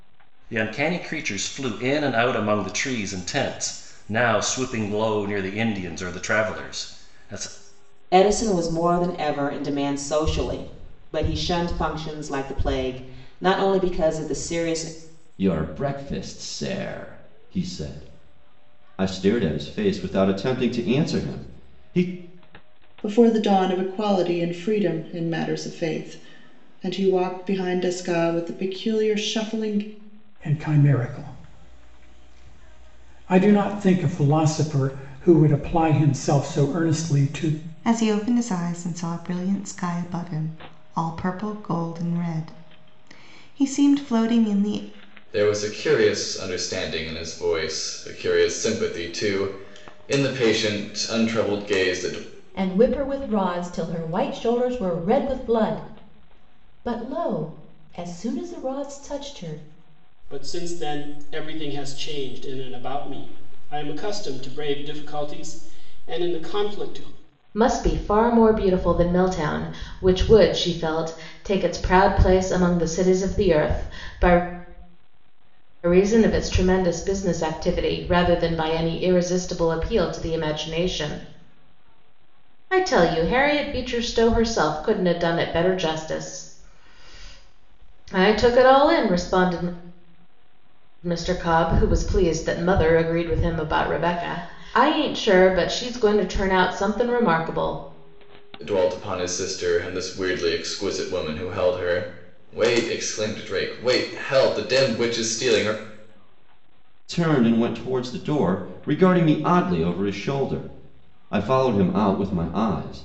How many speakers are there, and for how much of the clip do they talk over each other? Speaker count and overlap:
ten, no overlap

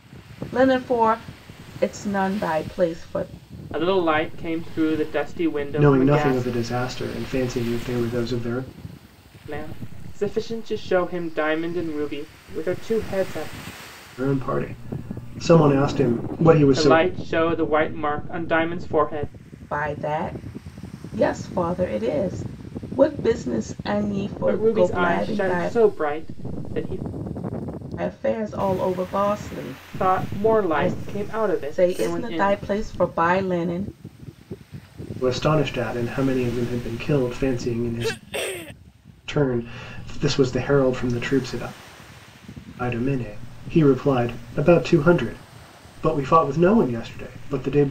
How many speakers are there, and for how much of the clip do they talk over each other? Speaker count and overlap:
three, about 9%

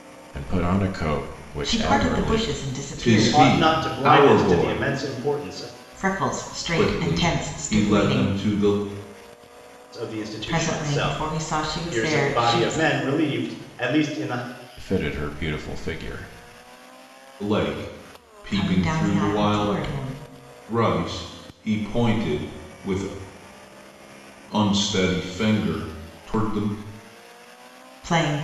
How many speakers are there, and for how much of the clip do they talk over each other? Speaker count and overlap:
four, about 29%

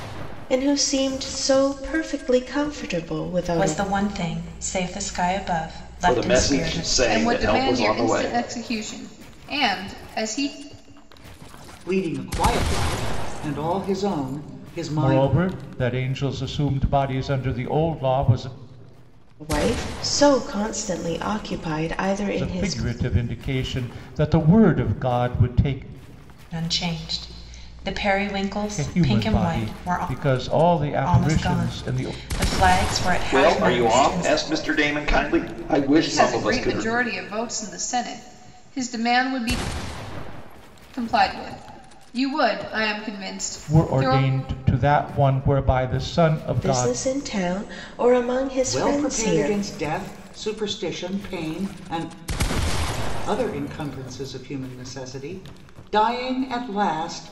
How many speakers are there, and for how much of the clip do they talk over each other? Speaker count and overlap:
six, about 17%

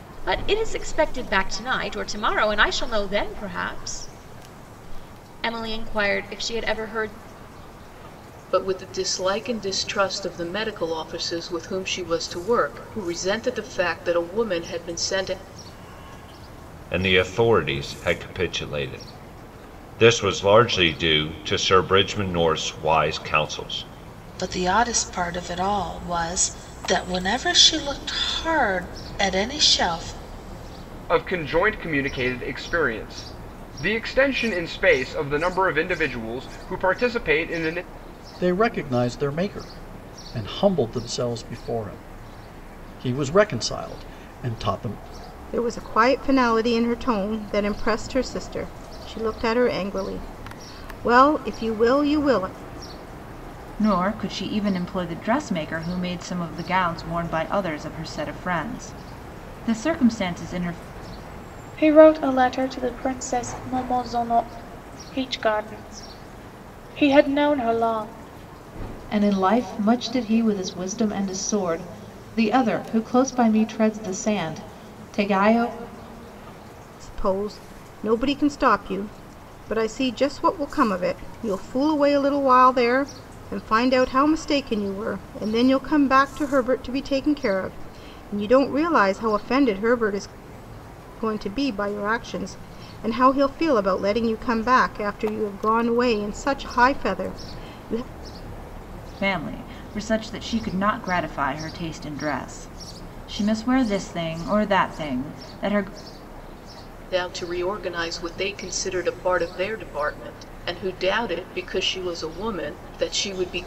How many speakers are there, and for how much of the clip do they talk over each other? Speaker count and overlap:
ten, no overlap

